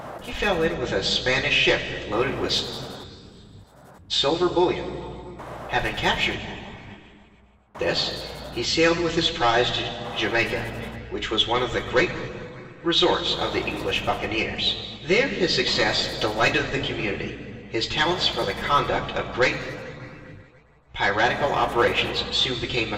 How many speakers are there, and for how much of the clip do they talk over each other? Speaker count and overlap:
1, no overlap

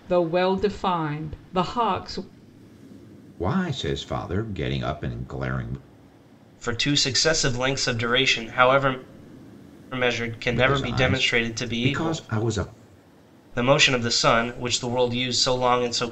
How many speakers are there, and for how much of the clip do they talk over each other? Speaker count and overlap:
3, about 11%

